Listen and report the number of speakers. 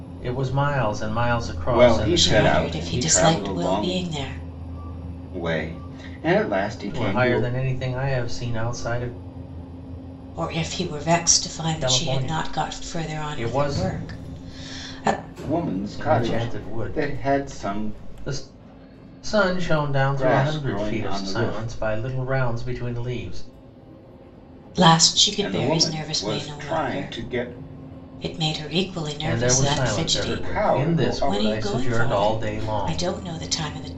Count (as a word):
three